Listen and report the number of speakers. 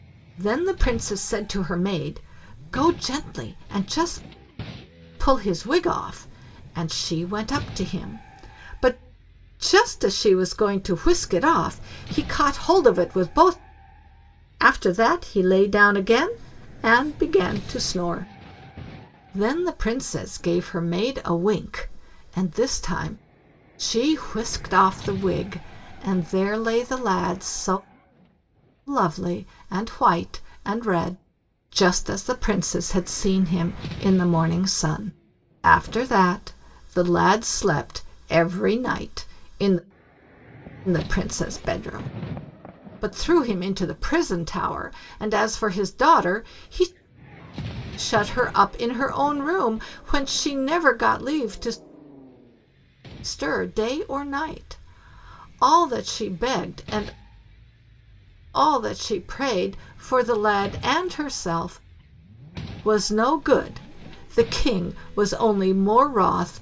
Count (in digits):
1